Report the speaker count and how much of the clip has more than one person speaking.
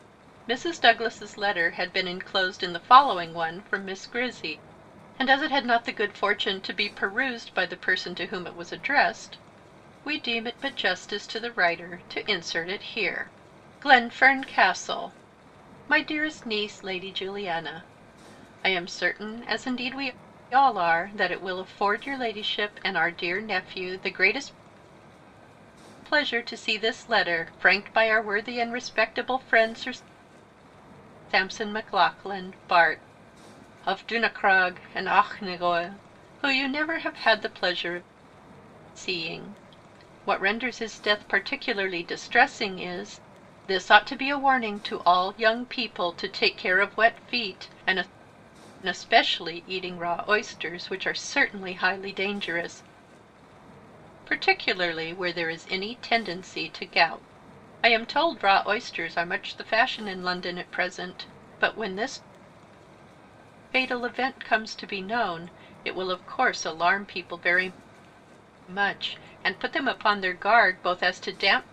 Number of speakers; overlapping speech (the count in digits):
1, no overlap